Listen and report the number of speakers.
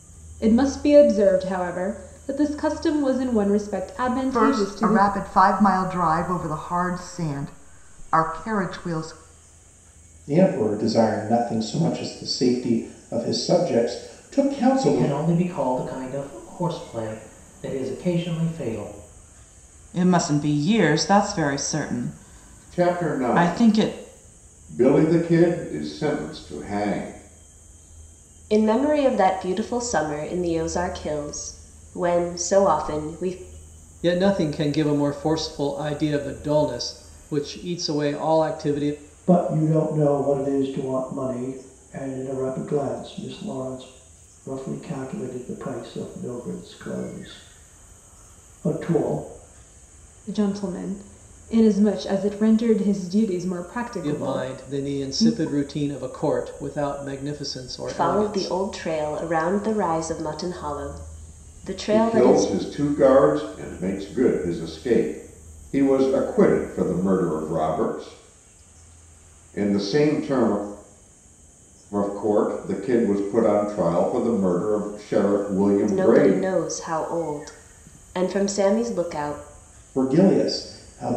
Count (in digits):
9